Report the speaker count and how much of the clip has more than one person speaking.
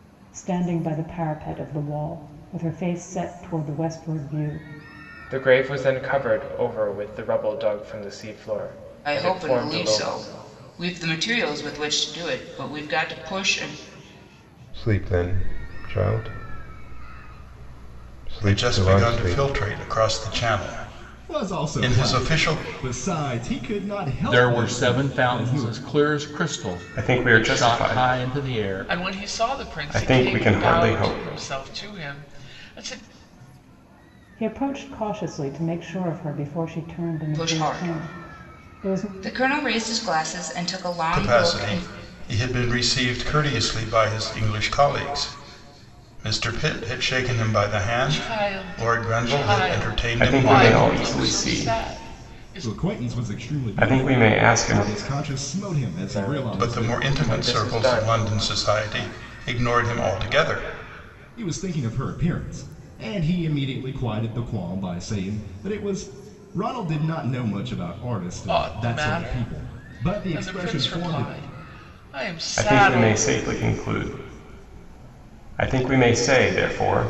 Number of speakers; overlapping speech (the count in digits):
9, about 32%